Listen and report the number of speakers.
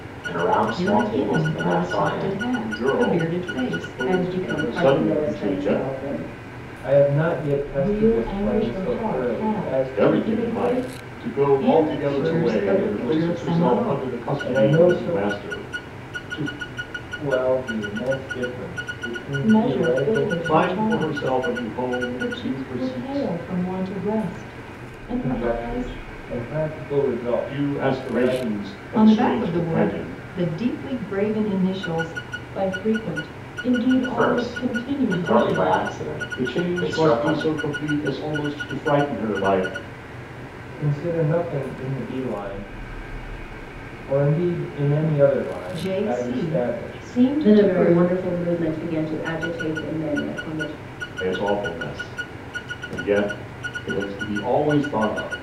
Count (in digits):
6